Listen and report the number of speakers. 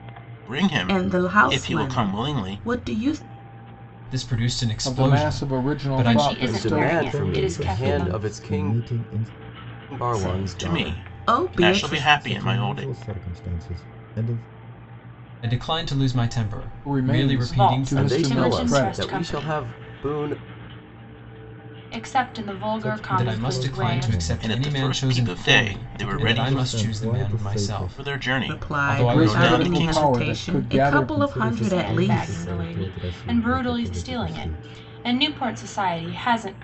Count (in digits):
7